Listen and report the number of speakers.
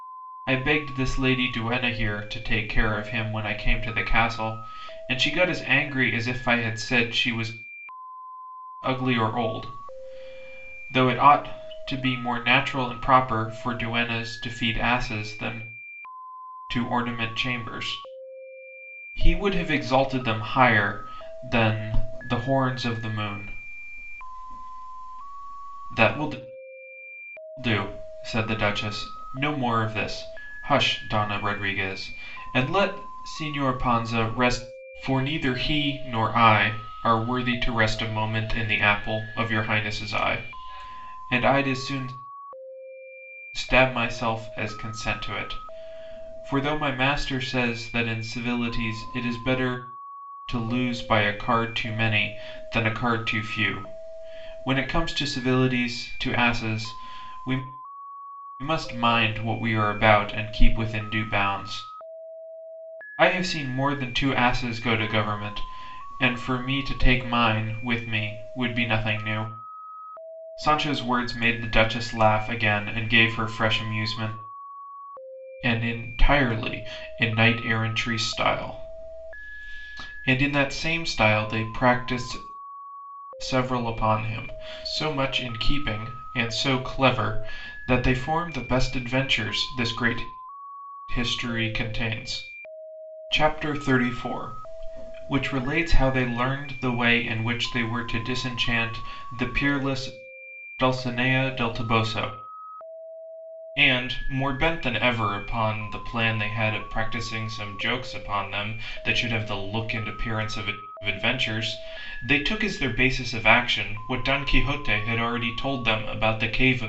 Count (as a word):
one